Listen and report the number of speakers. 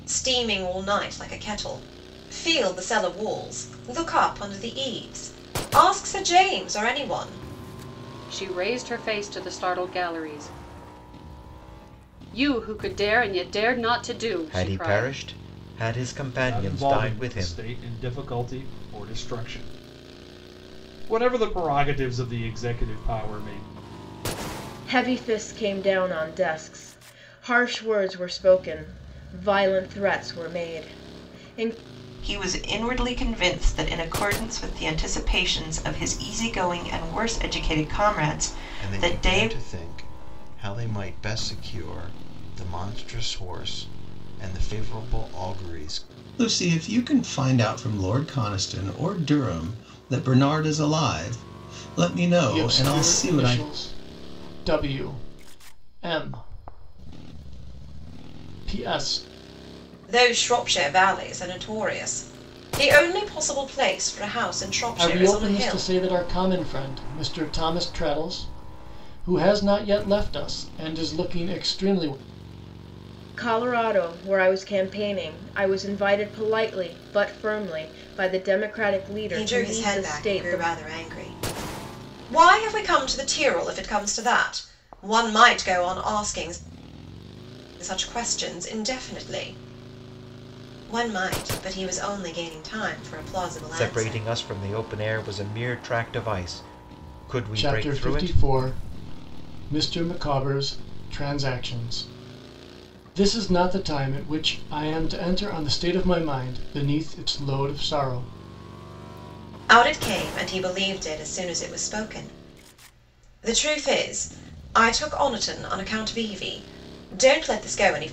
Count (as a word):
nine